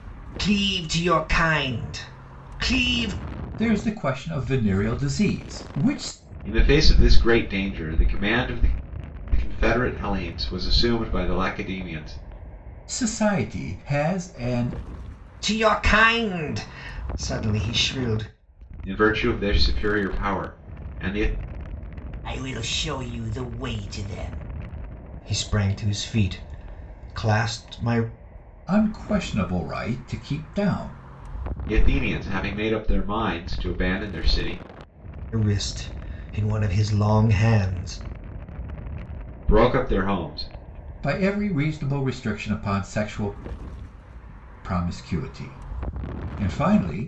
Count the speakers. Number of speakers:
3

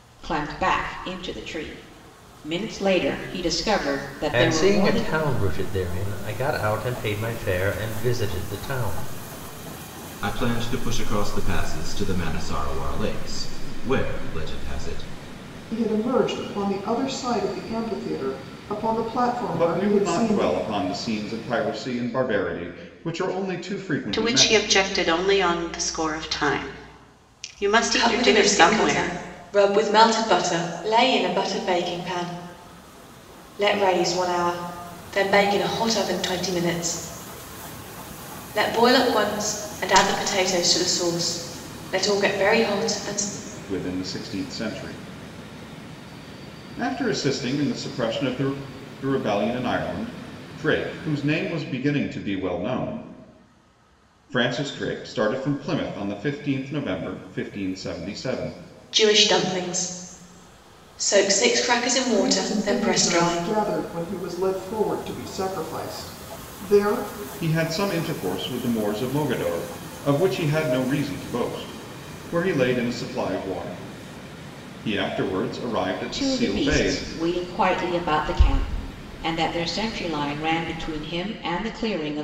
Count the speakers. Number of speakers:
7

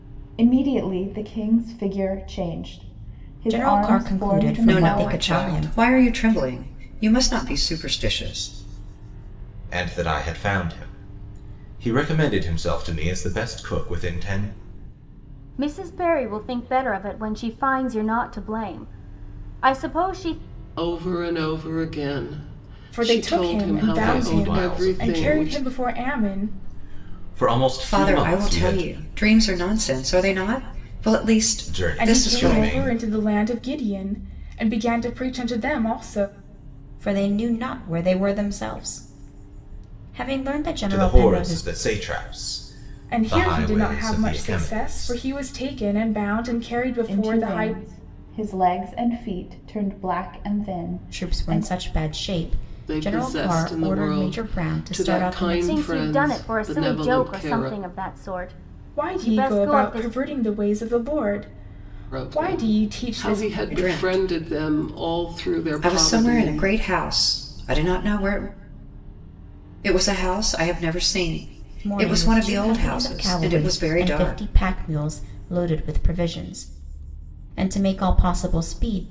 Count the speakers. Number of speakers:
7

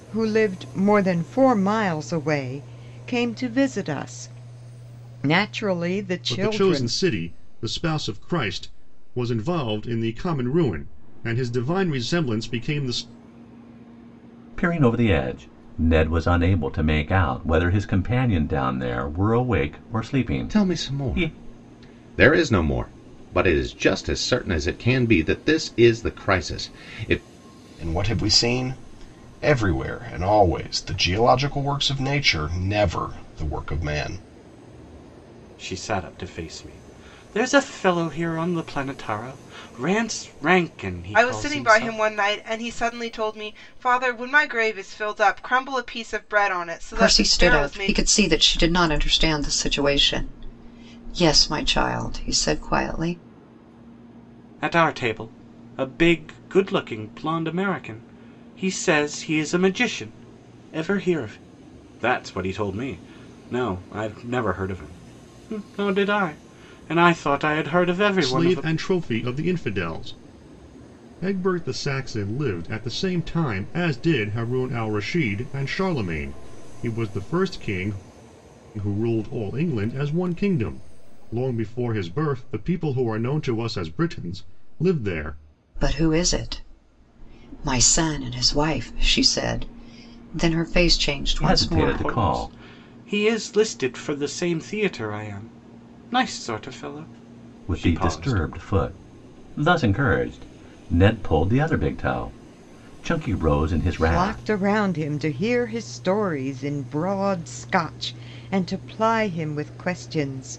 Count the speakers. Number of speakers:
8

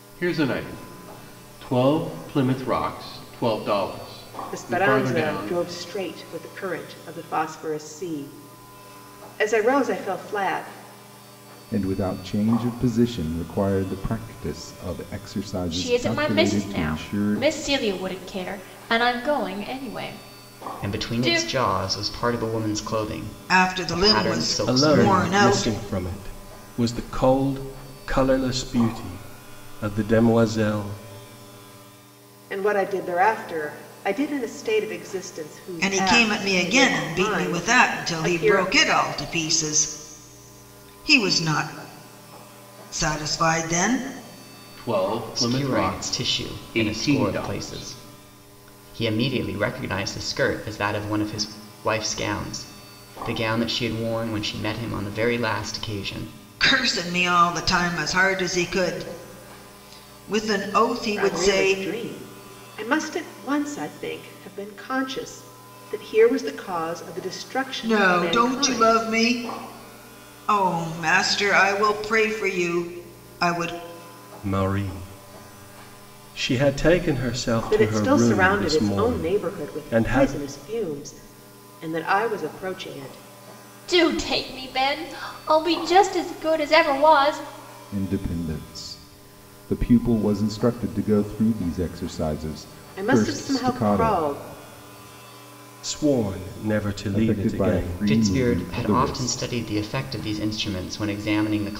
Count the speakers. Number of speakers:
7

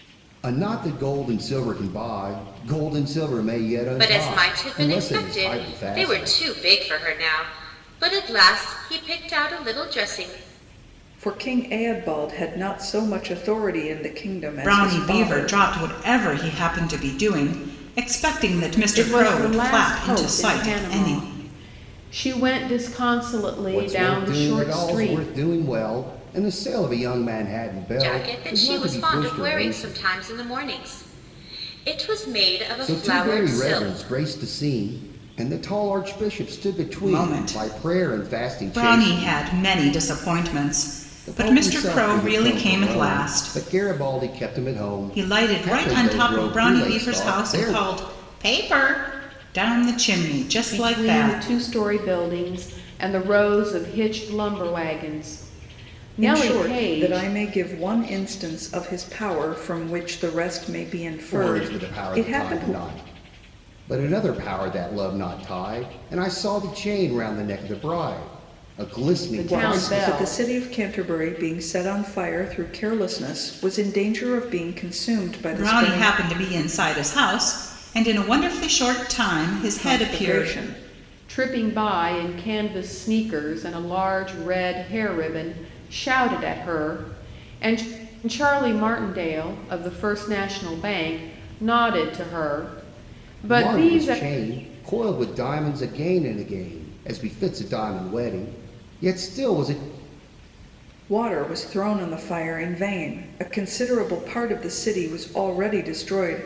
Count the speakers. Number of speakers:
5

